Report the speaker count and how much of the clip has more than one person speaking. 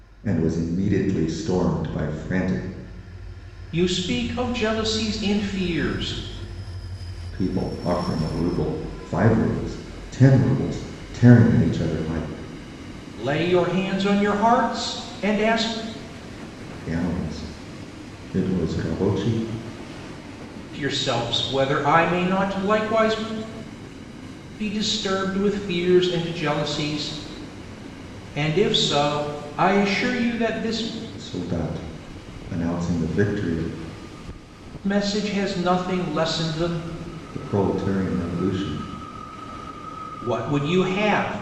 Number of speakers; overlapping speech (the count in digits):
2, no overlap